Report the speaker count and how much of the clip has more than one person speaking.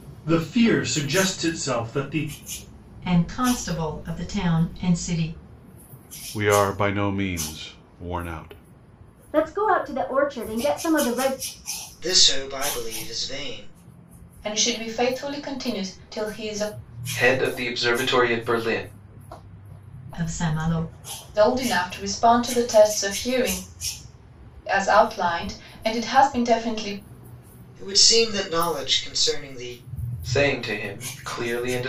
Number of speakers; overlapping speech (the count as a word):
seven, no overlap